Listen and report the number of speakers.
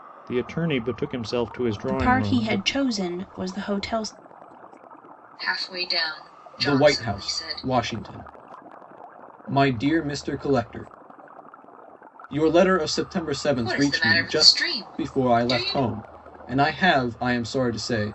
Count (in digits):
4